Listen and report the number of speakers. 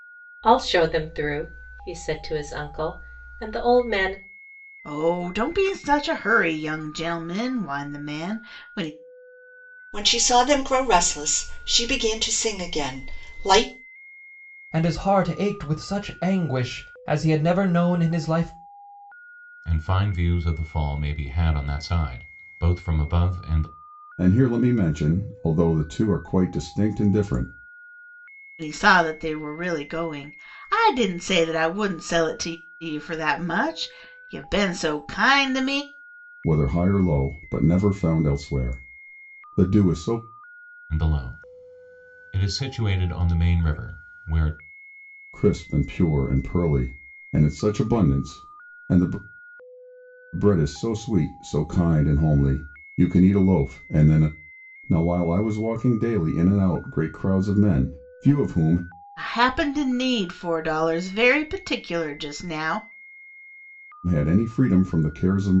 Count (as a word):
six